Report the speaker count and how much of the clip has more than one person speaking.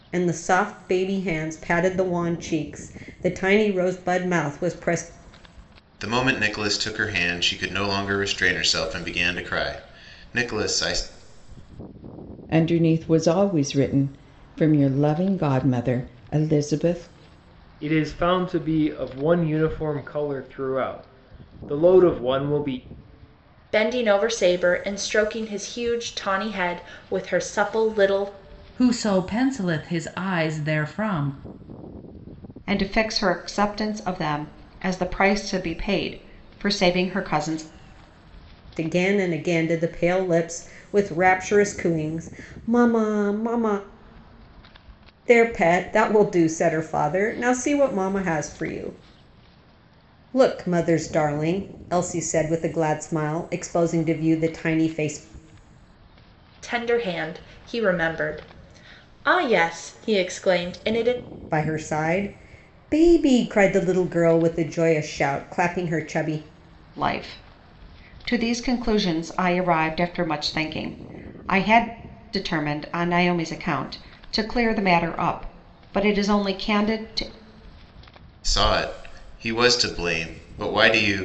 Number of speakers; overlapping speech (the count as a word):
seven, no overlap